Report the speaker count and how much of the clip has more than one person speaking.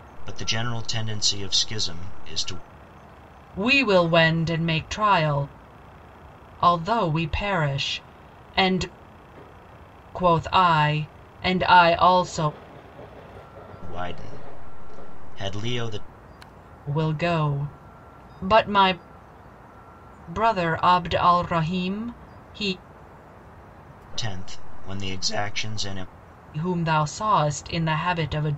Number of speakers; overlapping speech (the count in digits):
2, no overlap